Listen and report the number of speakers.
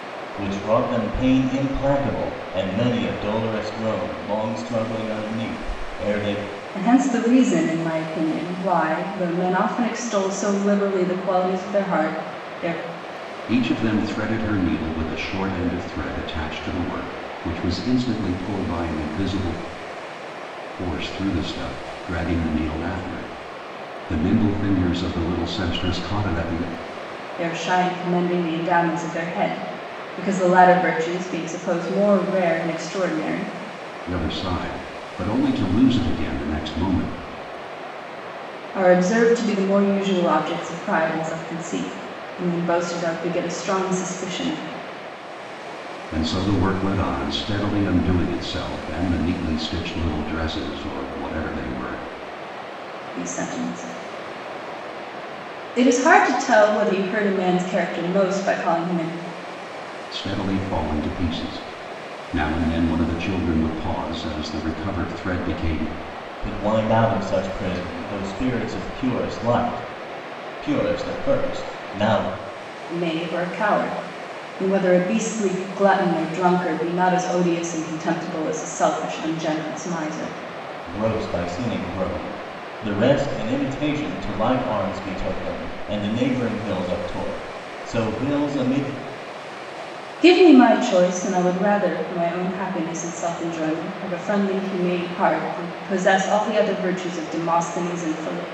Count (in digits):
3